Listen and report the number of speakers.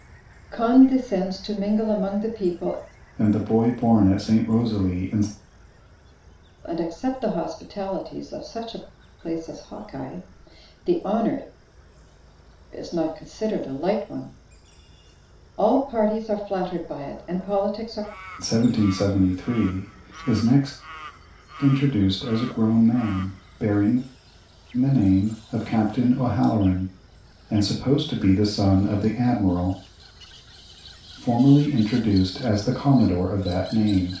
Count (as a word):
two